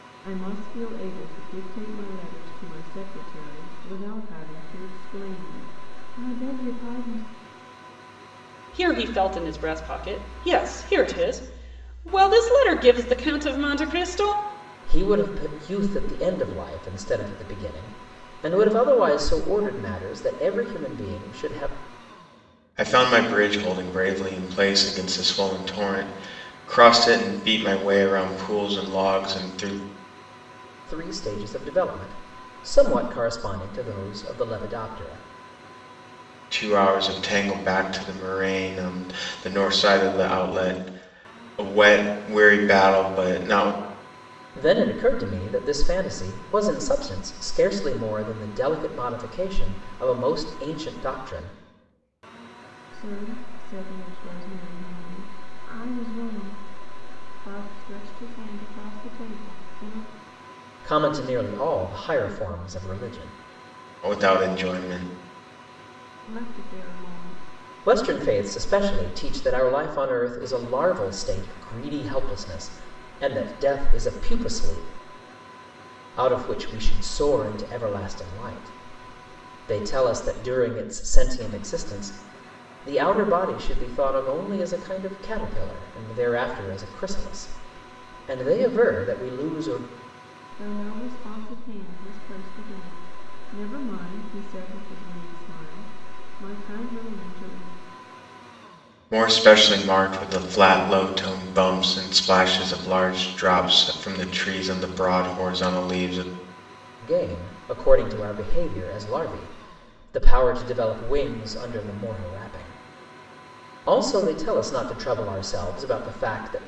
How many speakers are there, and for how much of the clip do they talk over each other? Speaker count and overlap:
4, no overlap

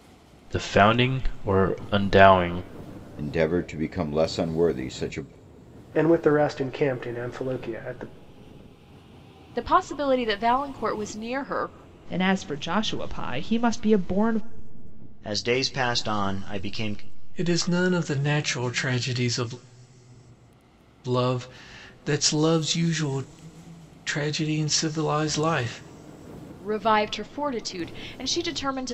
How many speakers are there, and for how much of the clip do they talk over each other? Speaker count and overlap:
7, no overlap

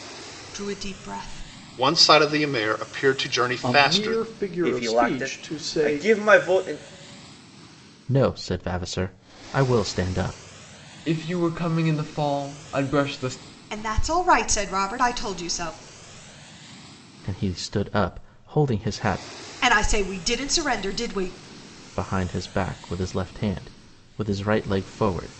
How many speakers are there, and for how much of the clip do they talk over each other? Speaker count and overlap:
6, about 8%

